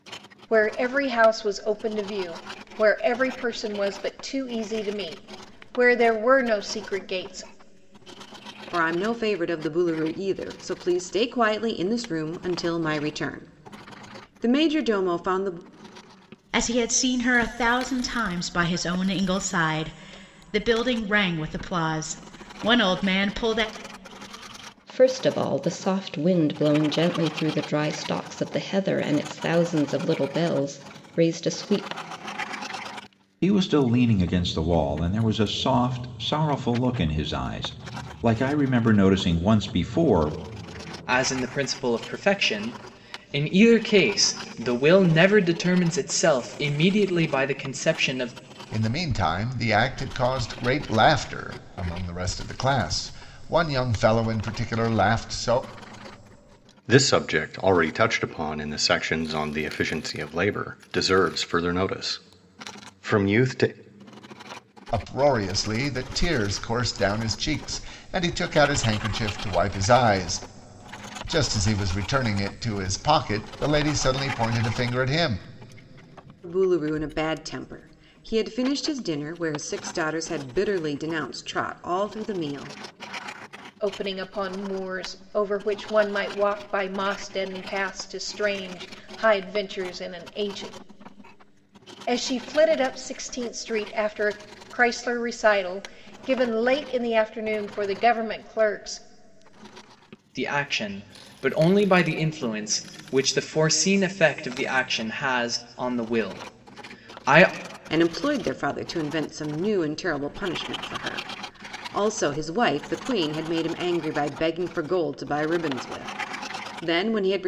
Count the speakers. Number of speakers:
8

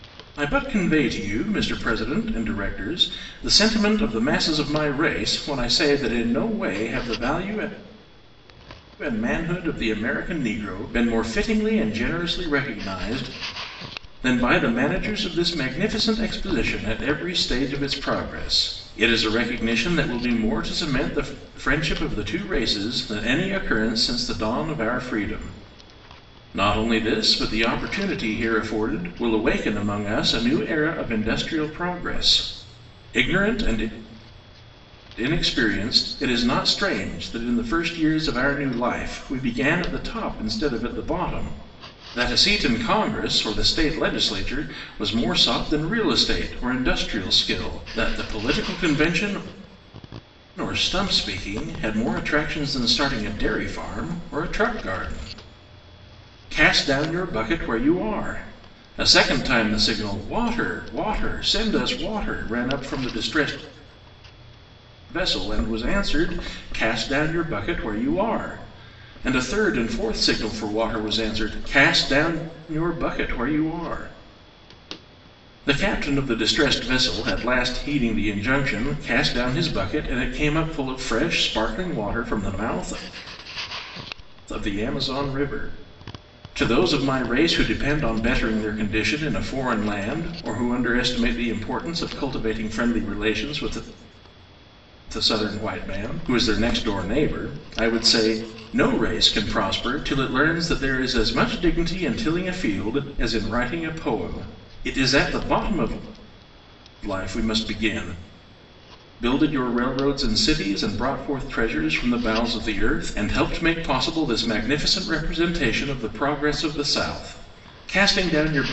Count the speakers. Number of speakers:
1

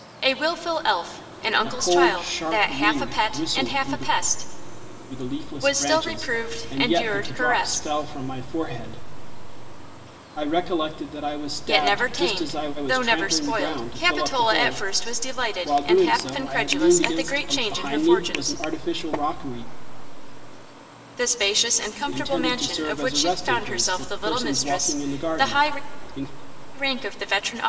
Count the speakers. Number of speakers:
2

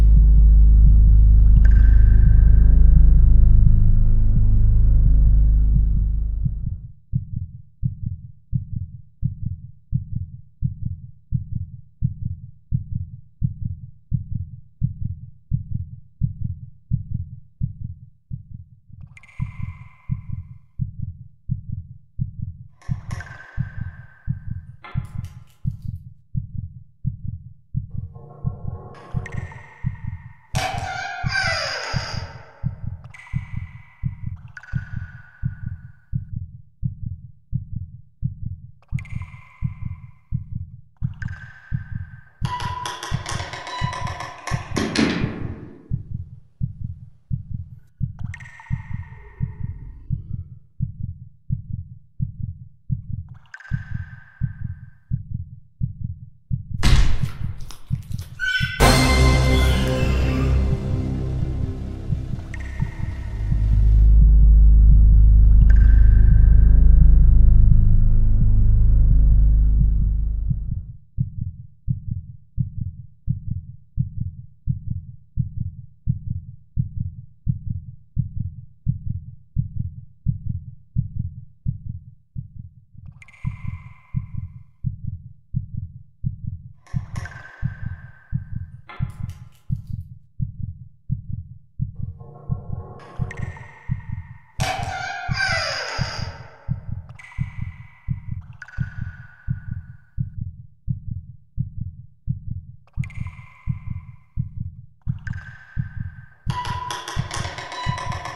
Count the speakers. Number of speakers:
0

